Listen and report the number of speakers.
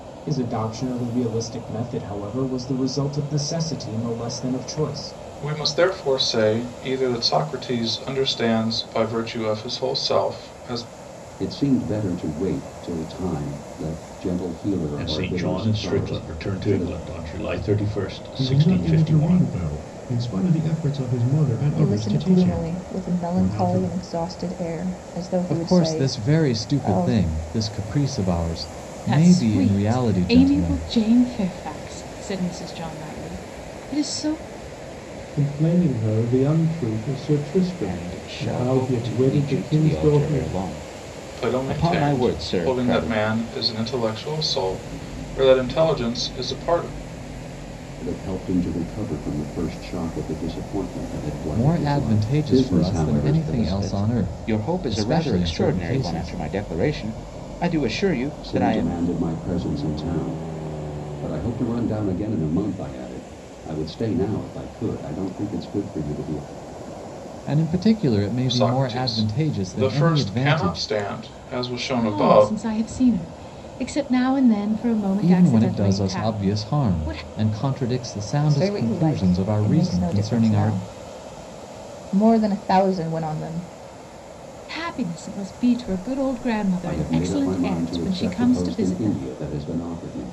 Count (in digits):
10